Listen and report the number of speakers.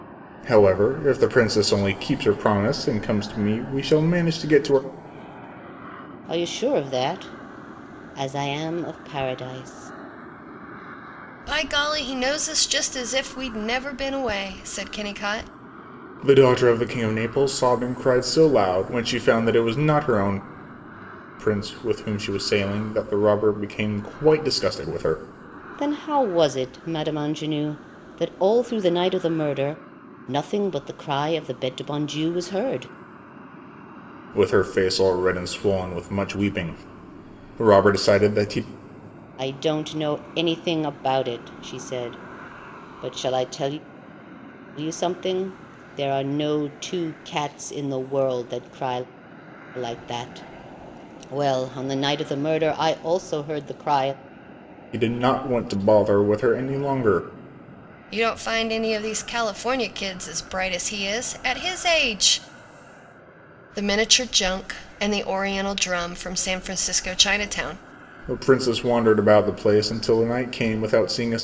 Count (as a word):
three